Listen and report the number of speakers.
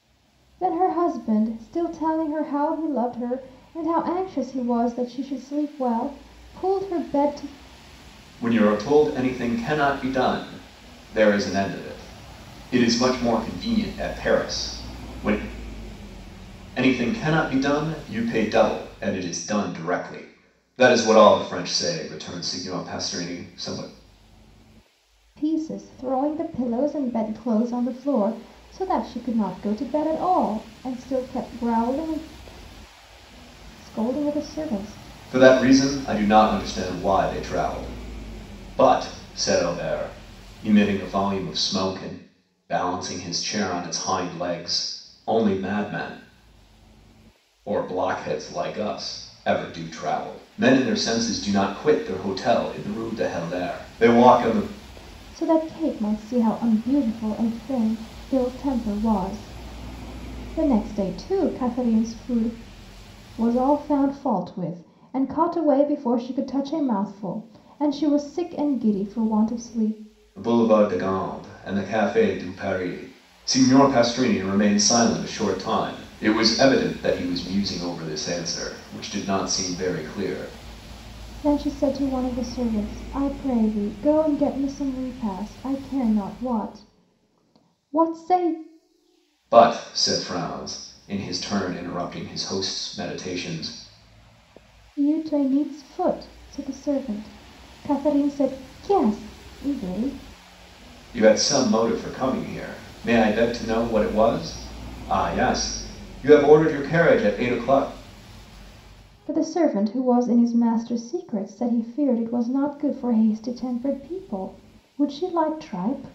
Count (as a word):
two